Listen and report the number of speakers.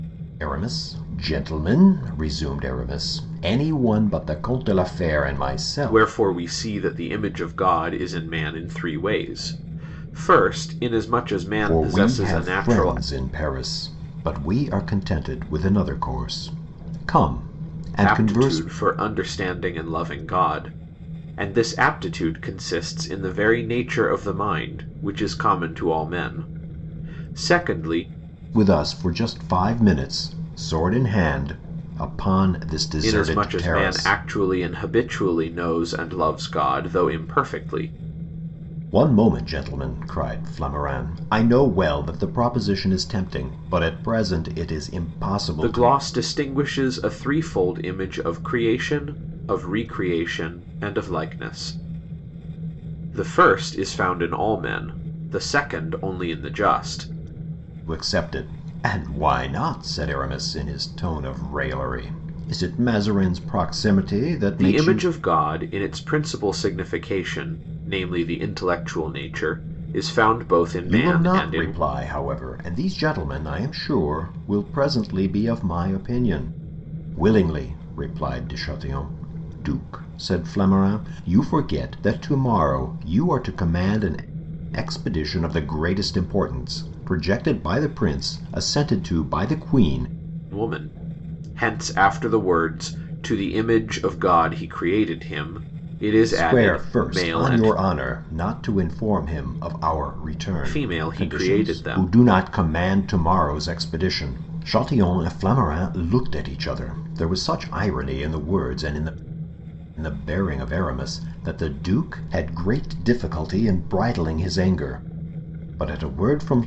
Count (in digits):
2